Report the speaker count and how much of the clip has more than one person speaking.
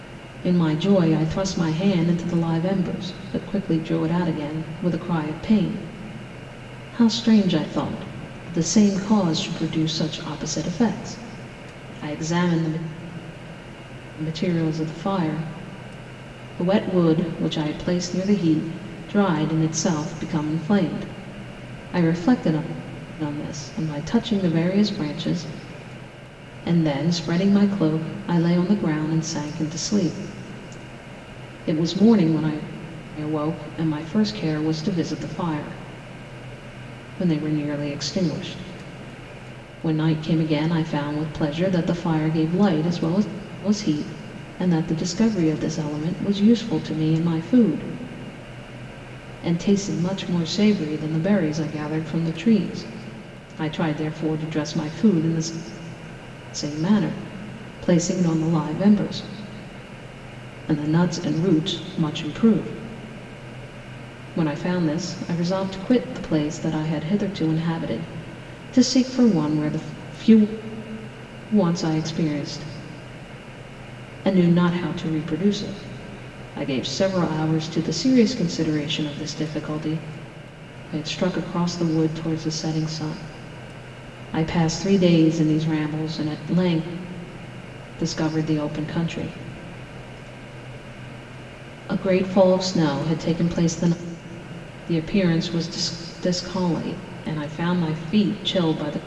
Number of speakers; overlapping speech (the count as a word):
one, no overlap